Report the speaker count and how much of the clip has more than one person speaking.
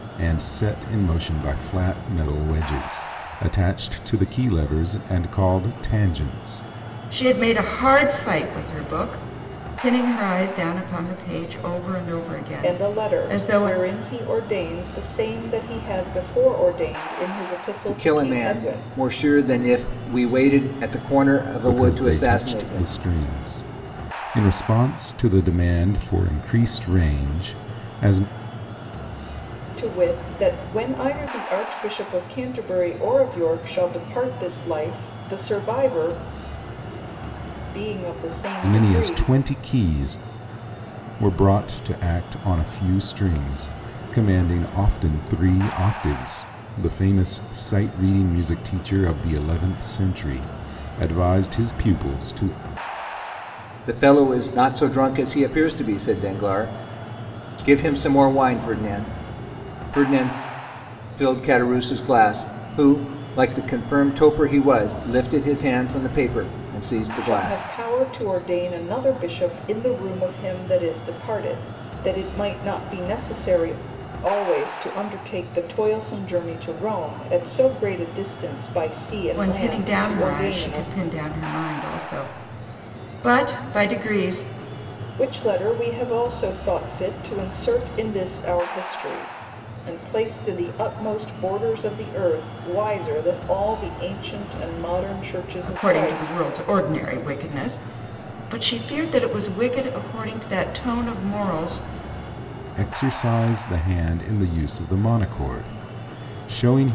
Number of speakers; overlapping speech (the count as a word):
four, about 7%